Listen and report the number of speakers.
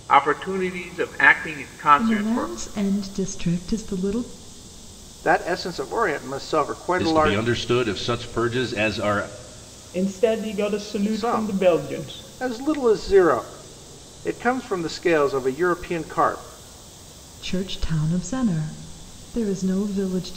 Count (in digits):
5